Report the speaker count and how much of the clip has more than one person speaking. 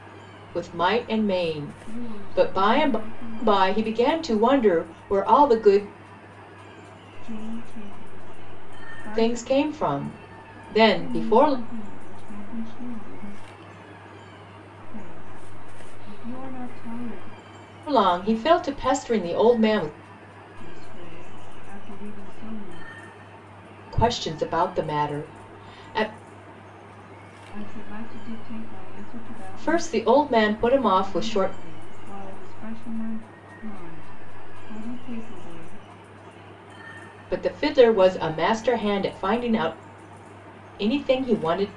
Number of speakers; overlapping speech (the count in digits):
2, about 8%